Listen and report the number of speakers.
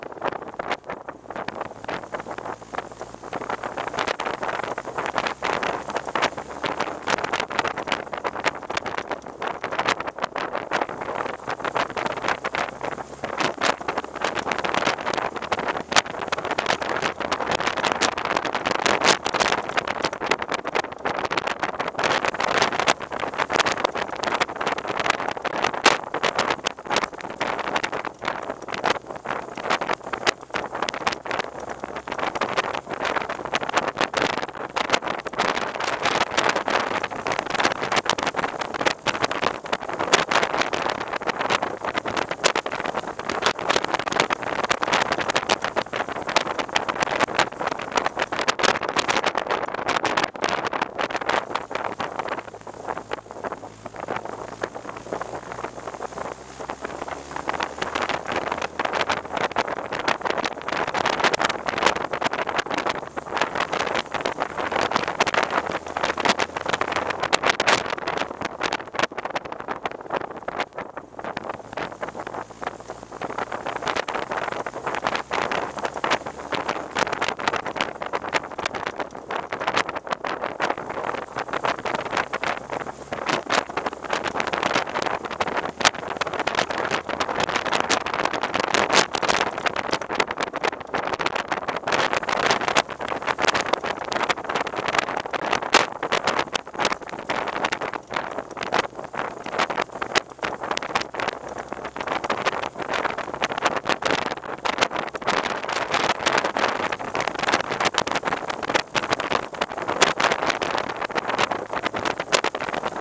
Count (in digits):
0